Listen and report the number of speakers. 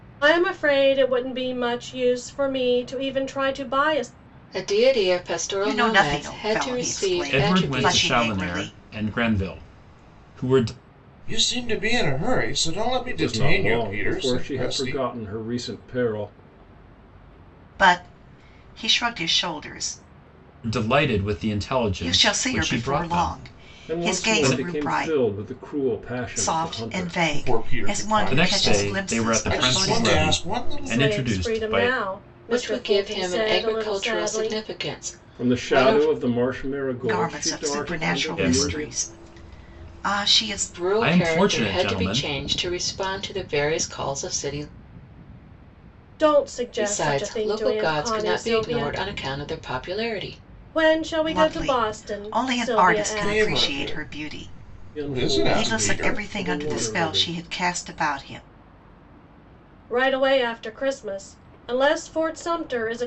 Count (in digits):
6